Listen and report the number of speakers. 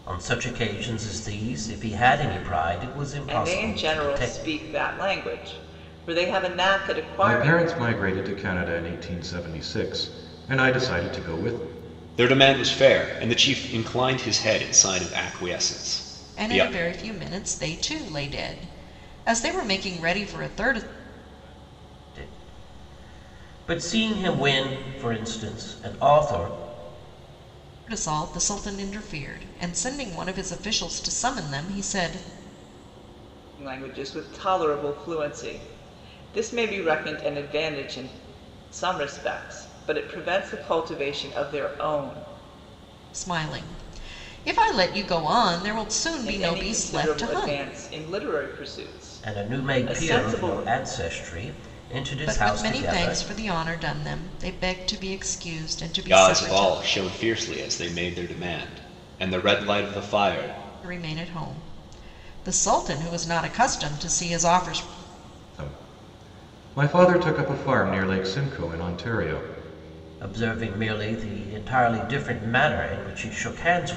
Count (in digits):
5